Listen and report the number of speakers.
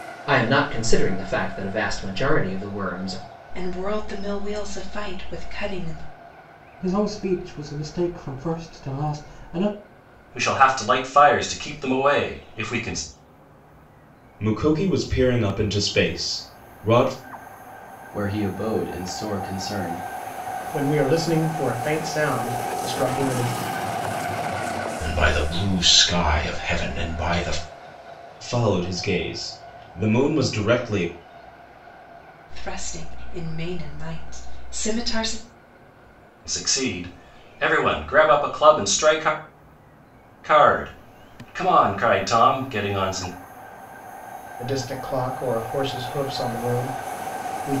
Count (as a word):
eight